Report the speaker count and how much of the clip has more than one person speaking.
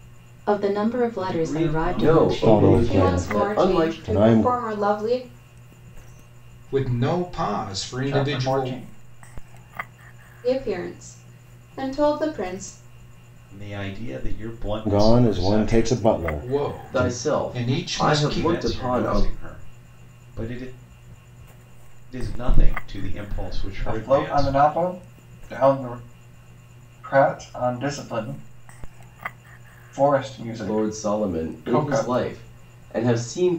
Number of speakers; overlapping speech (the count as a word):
seven, about 31%